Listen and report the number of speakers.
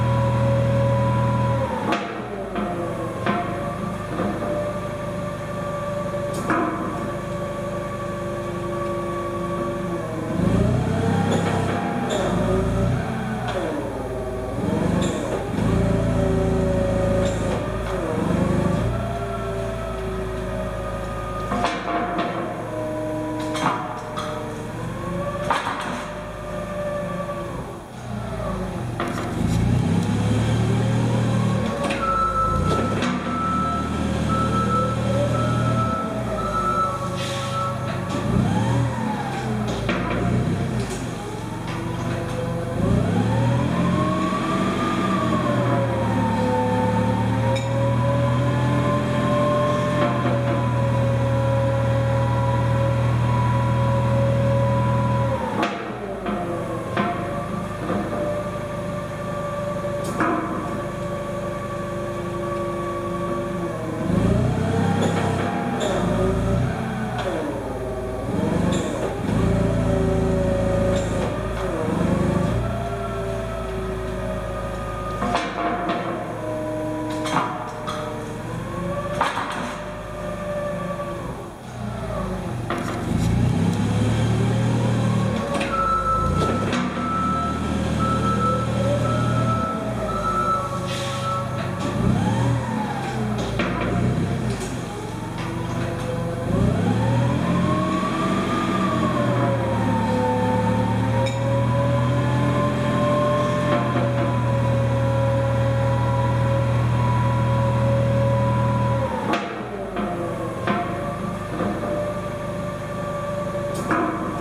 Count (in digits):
0